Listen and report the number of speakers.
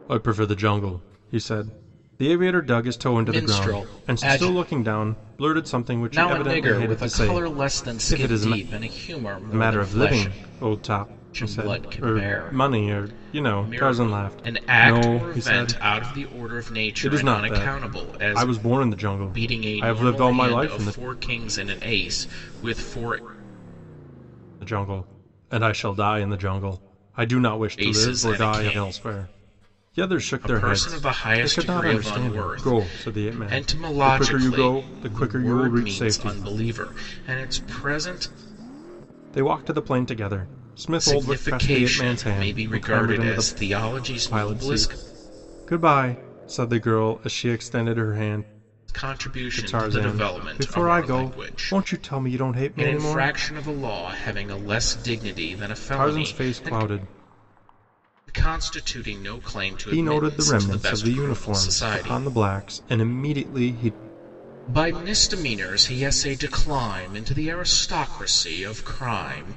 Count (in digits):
2